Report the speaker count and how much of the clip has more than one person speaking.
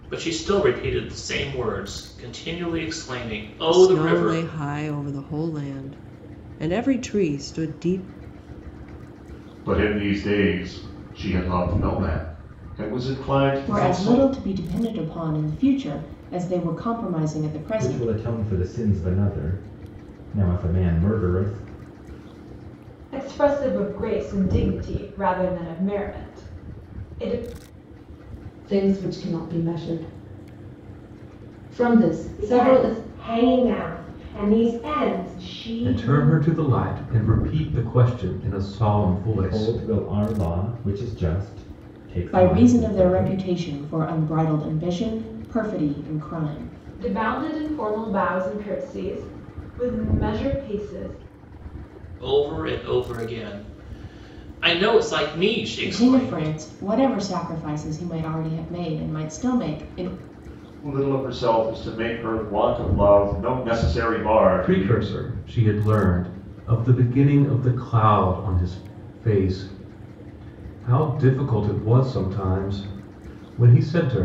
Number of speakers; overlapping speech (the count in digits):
9, about 8%